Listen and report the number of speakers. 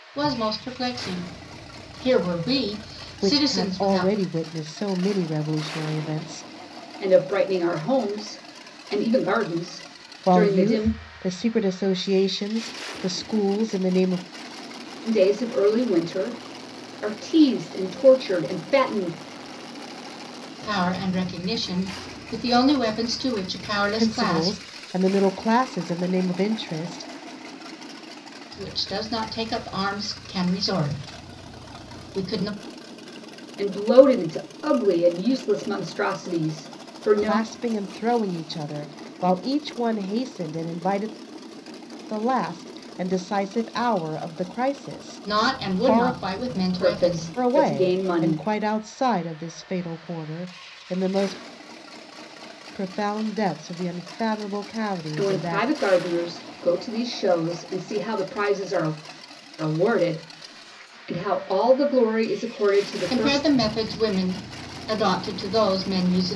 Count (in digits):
3